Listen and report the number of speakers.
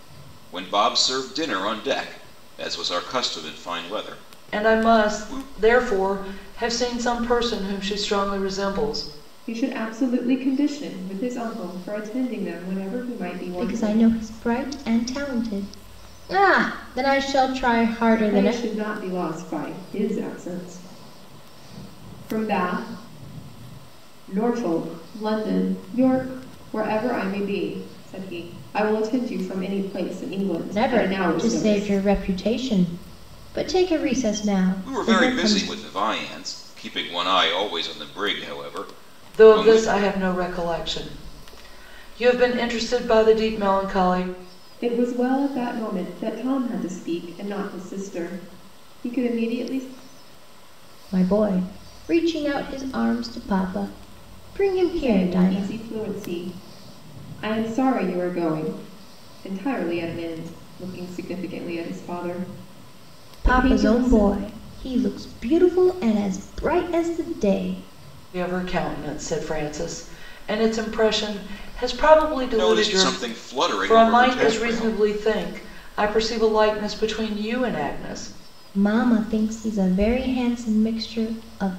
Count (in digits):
4